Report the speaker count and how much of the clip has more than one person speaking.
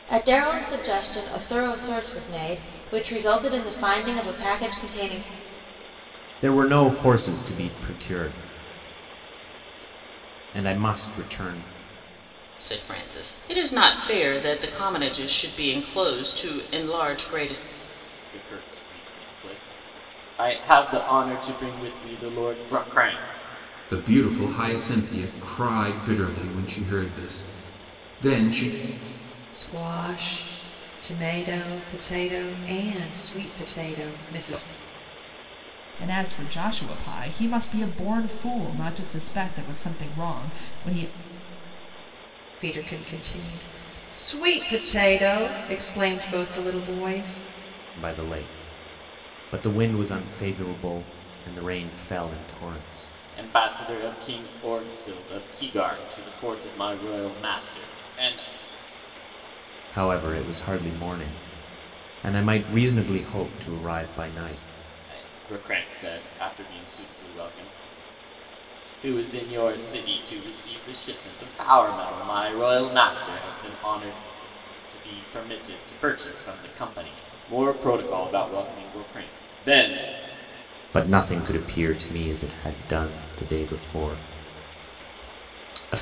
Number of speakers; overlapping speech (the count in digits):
7, no overlap